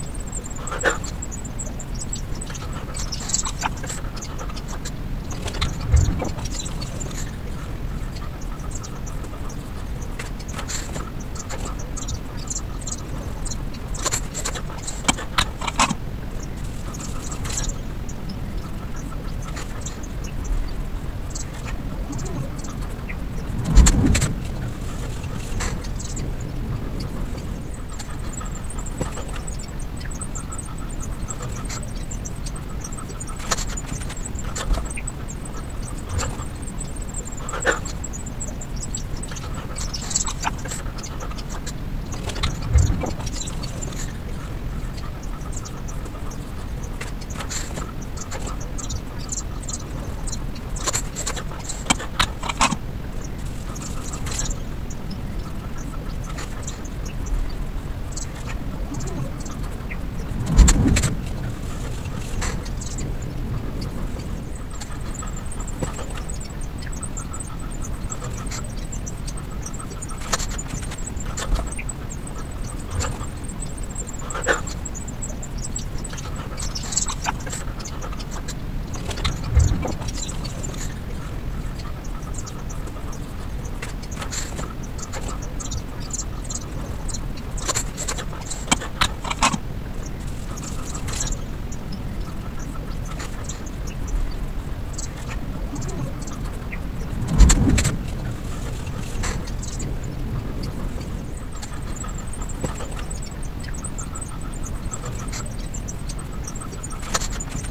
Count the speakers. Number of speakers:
zero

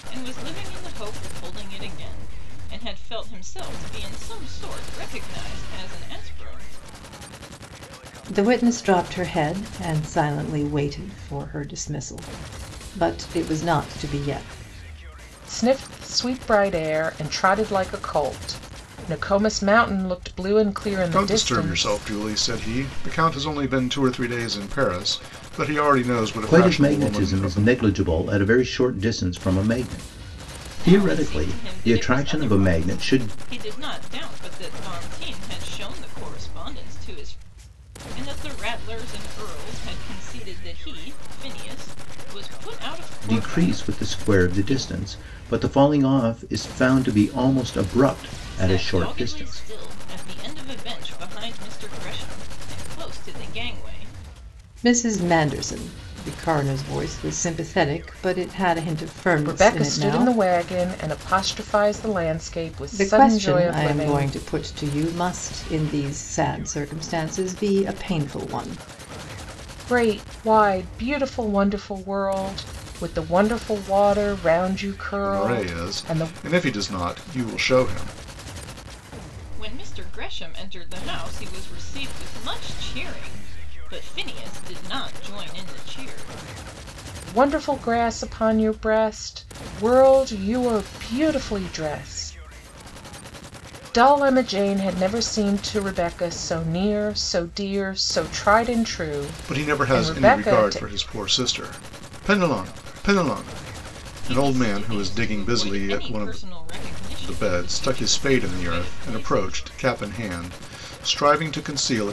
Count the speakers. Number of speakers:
five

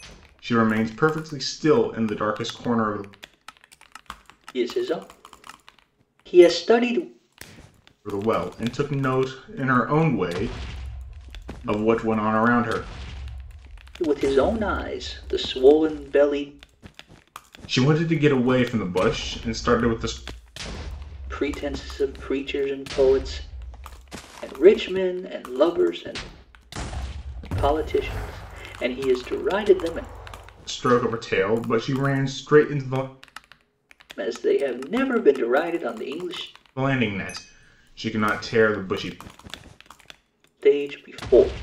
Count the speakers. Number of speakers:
two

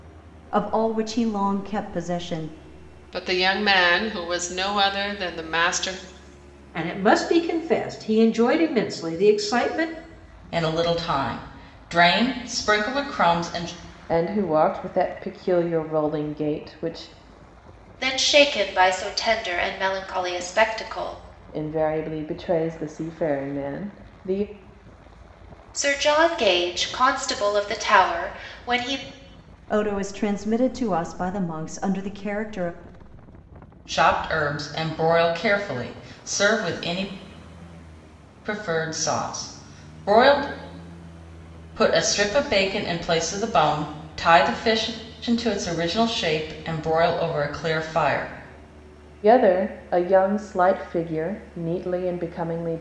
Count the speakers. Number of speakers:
six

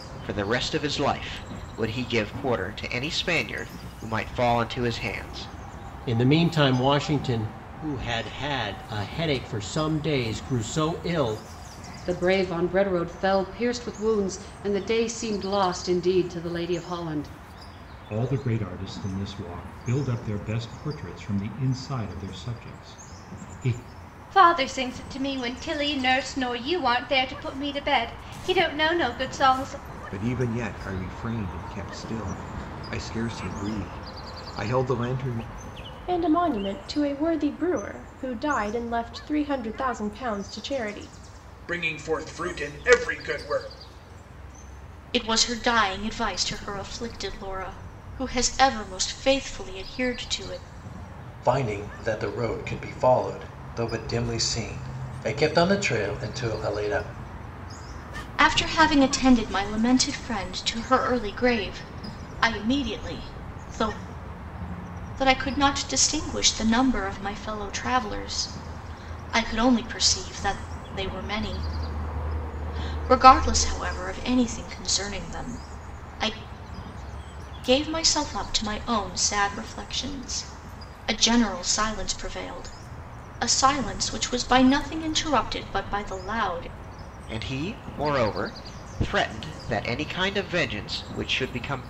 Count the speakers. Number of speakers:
ten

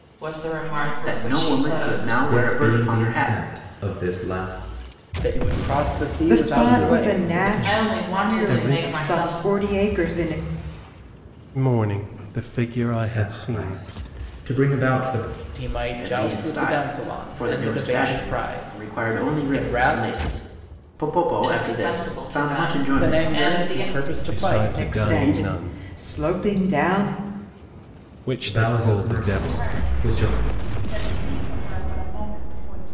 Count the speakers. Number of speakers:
seven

